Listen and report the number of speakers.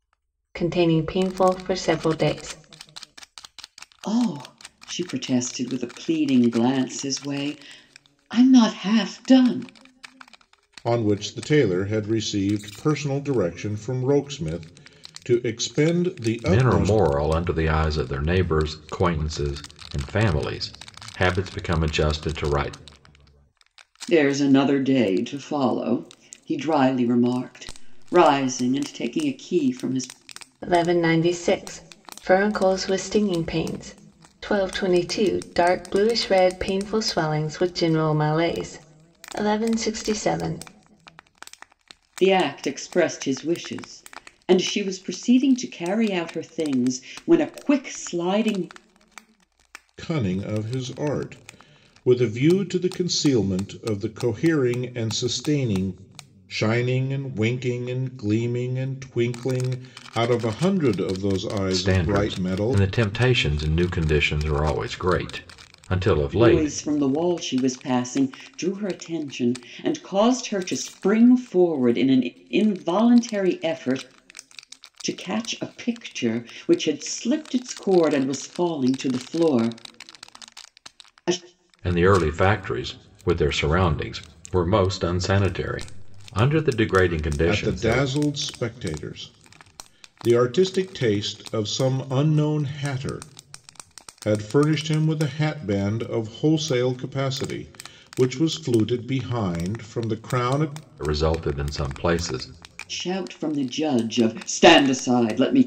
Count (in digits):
4